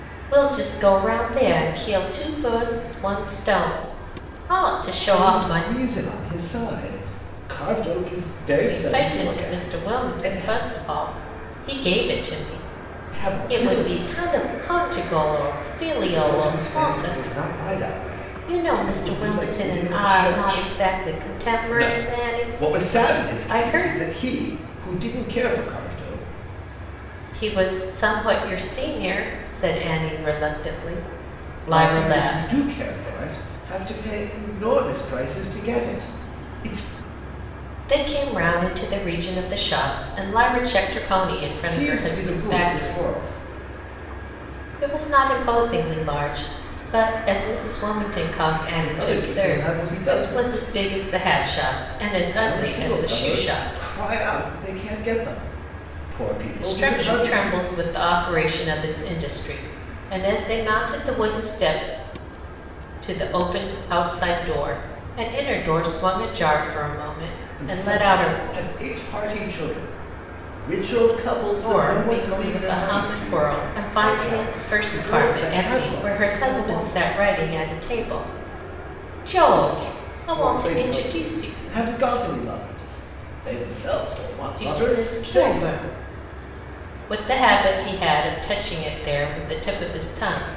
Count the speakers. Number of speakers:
two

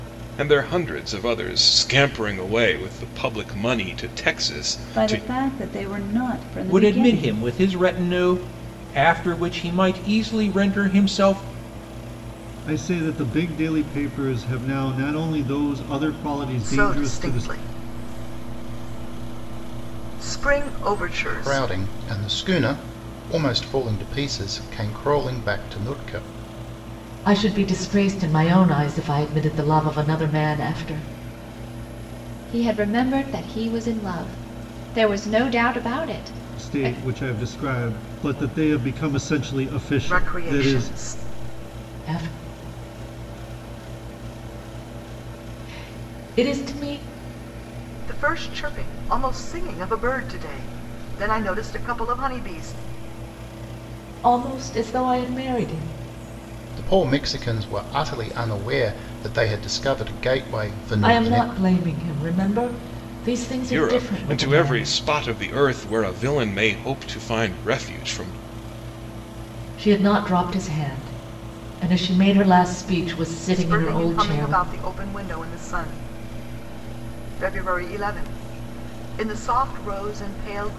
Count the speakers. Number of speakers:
eight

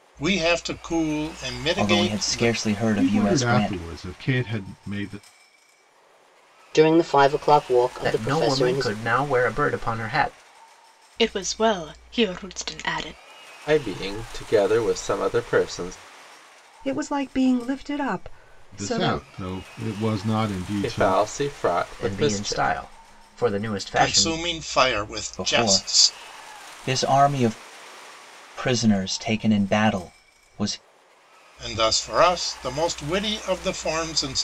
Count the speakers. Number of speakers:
eight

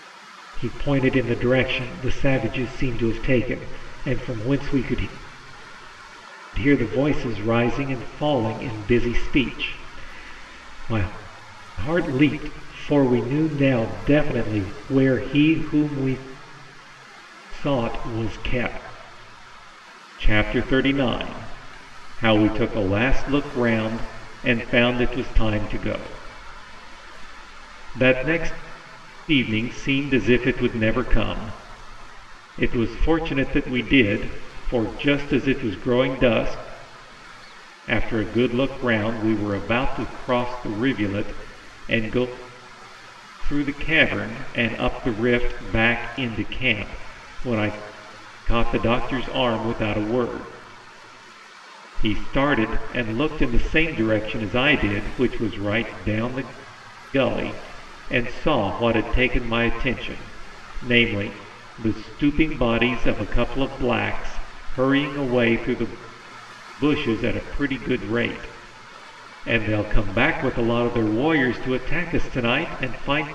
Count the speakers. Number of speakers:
one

